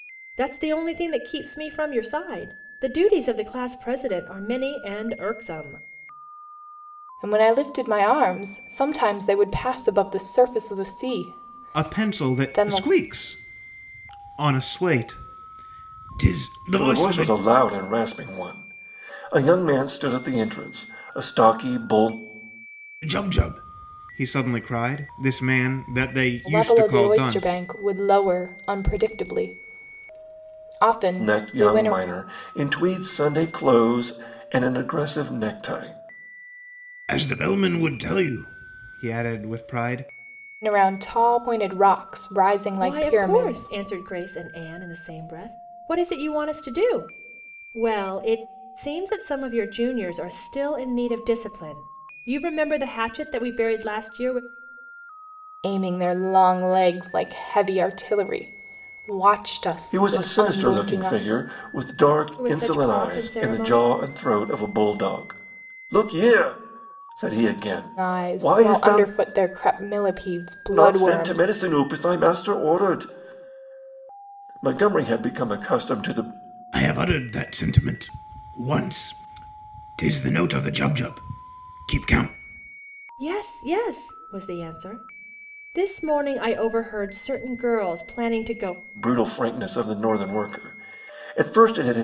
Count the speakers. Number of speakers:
four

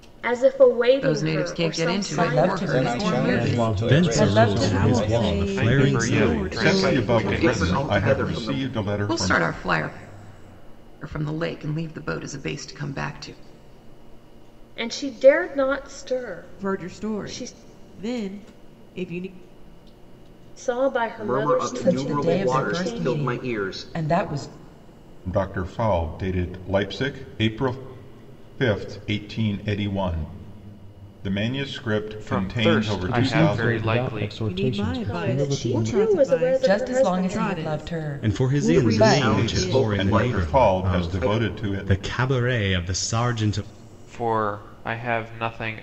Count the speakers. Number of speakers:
ten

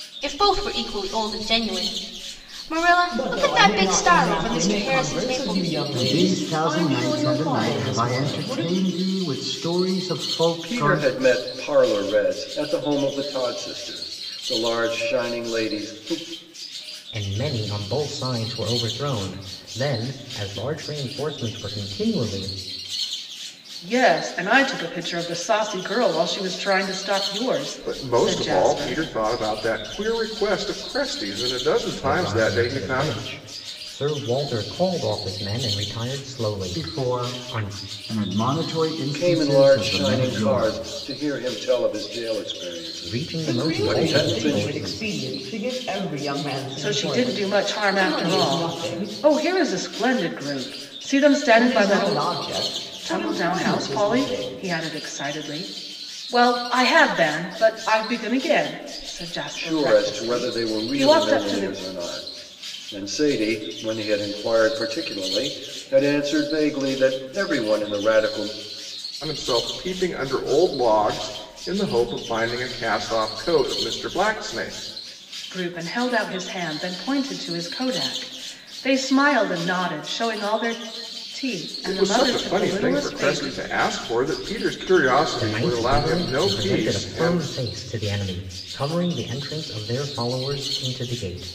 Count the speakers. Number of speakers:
seven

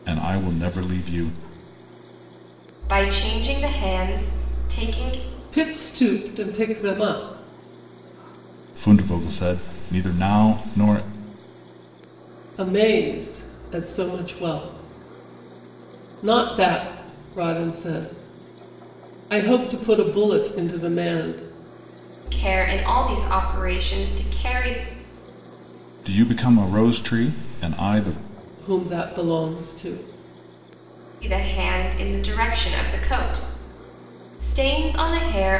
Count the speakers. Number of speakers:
three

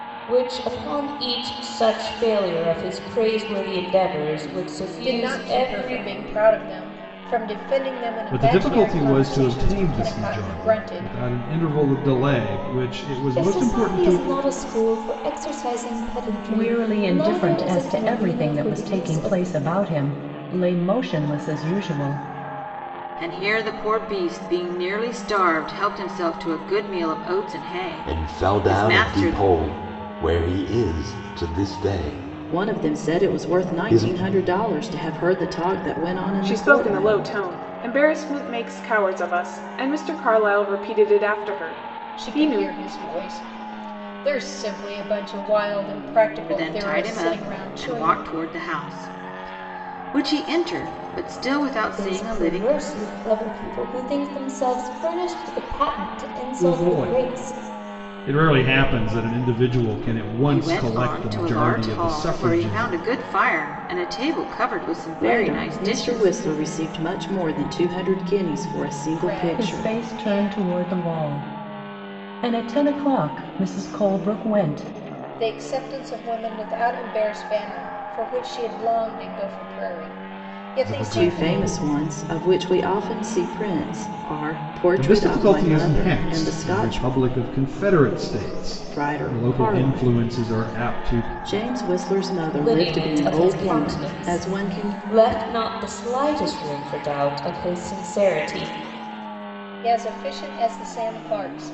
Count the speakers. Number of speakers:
nine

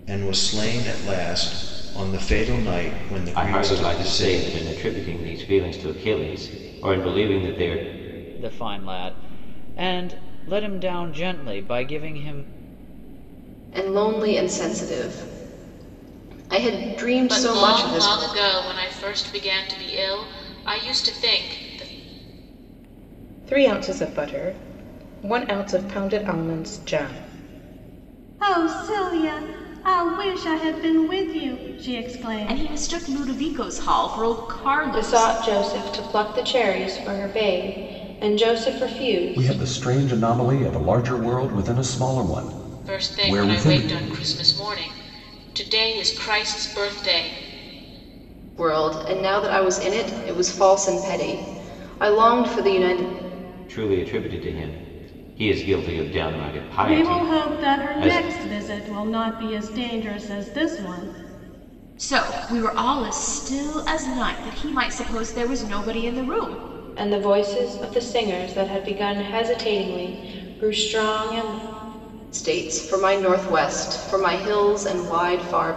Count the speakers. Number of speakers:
ten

